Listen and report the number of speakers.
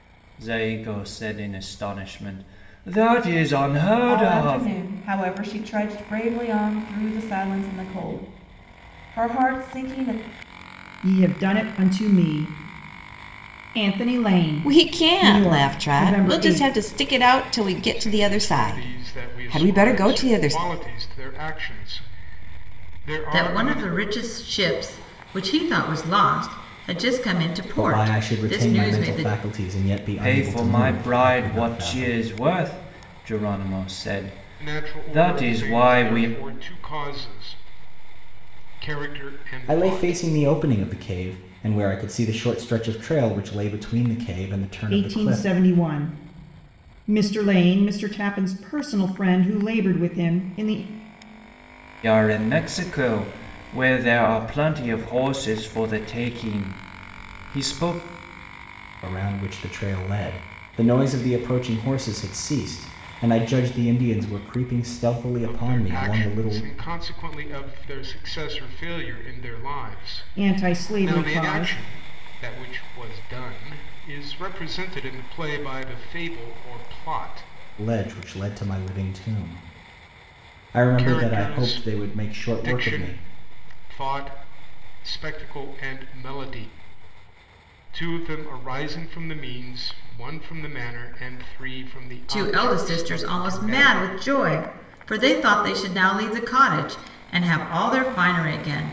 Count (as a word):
seven